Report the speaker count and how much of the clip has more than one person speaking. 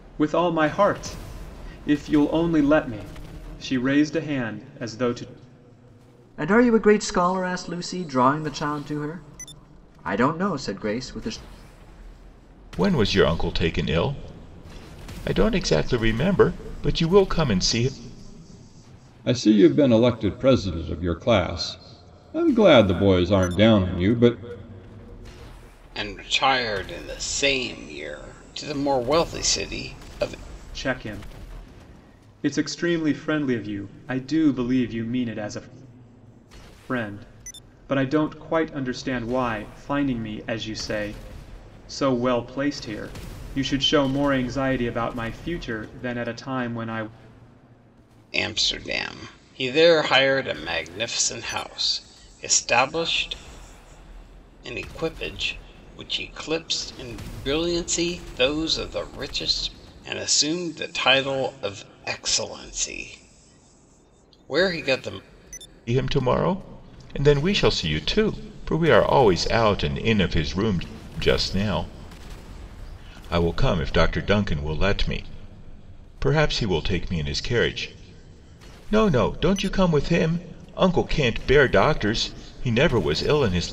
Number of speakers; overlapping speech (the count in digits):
5, no overlap